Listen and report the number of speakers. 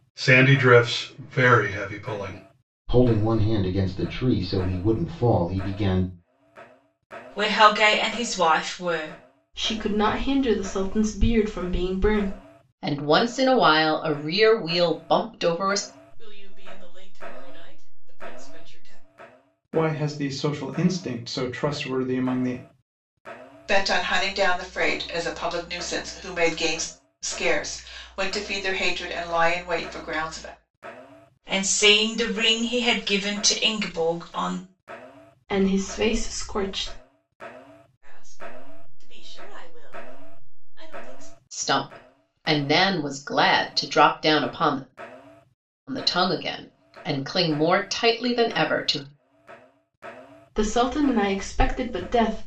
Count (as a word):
eight